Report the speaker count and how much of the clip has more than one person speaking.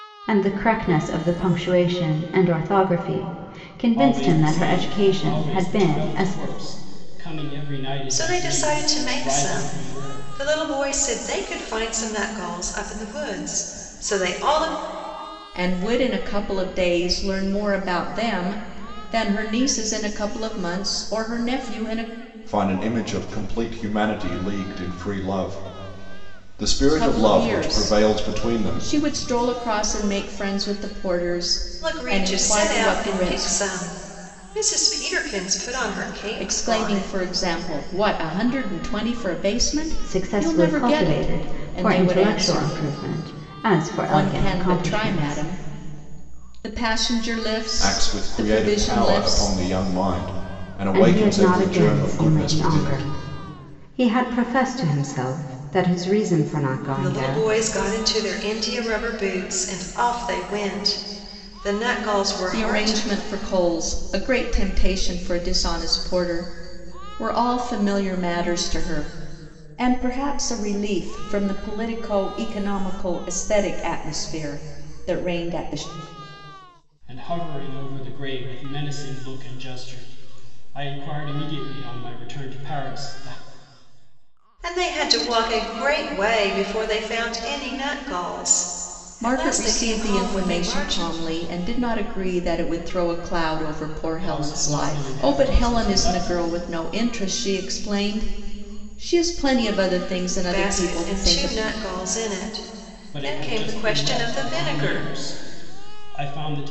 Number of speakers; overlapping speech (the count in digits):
5, about 24%